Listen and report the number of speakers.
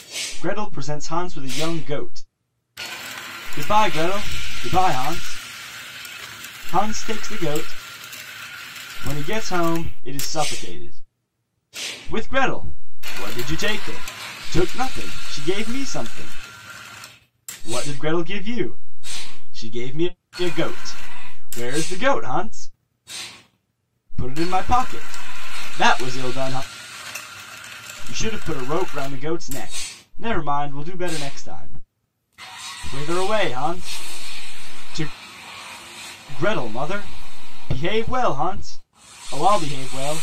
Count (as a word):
one